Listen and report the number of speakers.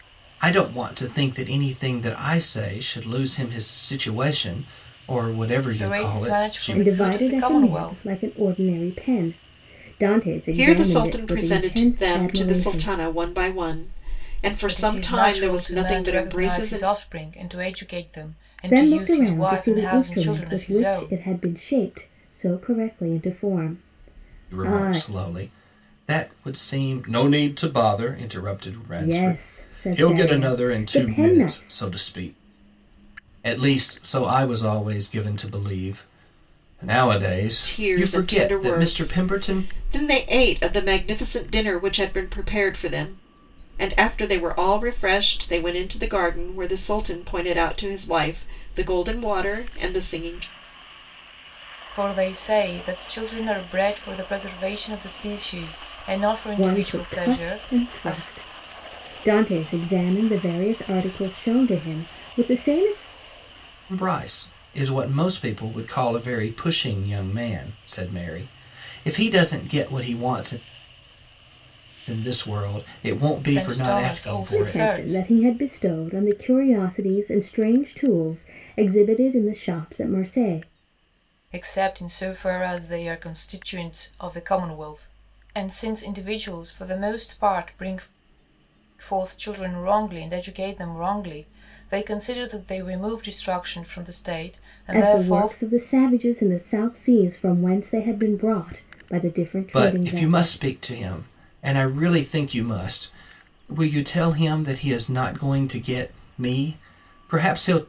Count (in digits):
4